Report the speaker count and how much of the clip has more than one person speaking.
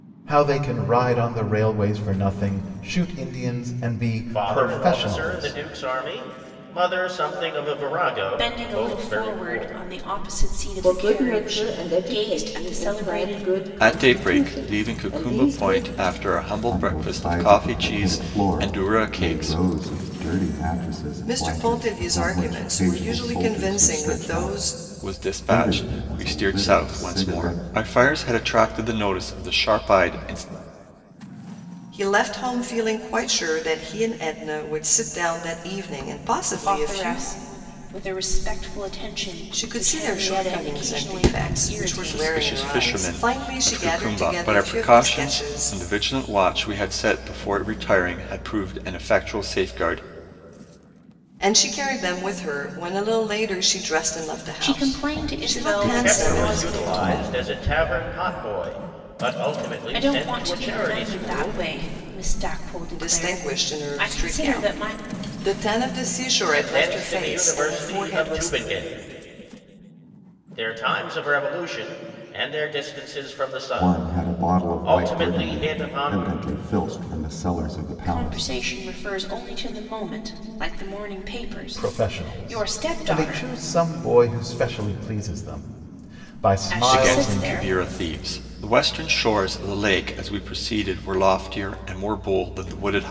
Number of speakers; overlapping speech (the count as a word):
seven, about 41%